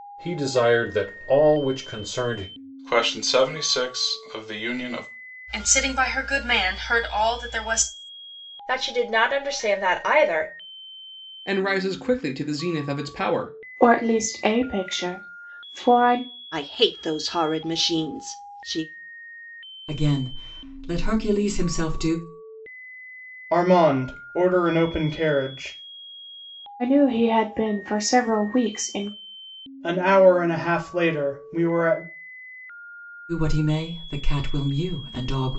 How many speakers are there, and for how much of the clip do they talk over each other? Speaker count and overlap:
9, no overlap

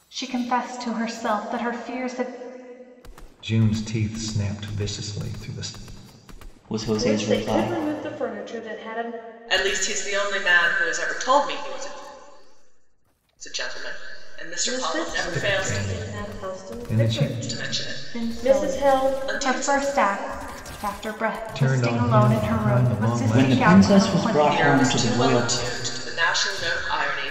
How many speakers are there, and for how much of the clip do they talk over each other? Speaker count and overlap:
5, about 36%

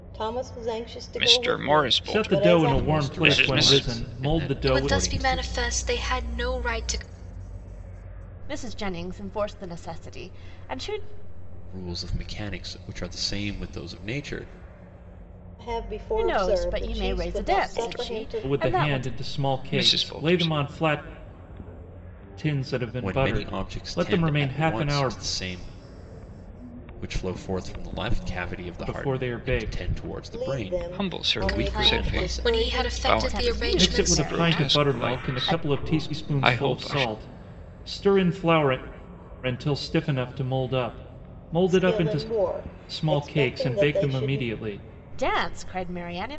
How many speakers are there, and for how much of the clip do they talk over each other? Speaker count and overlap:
6, about 45%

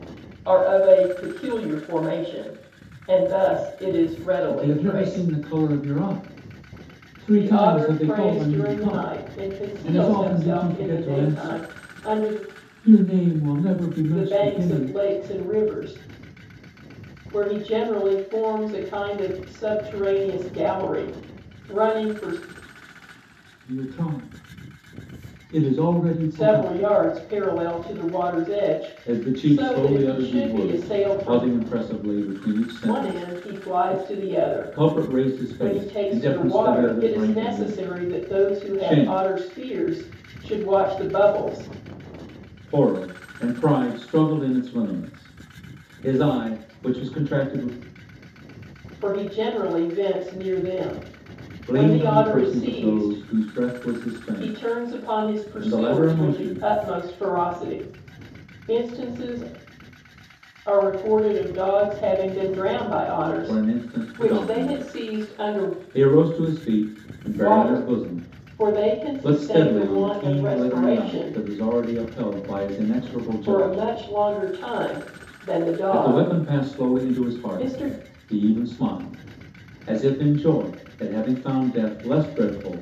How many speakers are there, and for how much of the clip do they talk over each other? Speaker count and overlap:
2, about 33%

